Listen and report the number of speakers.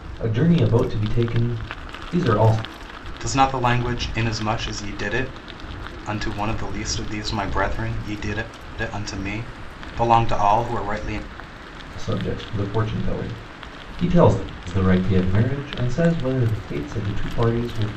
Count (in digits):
2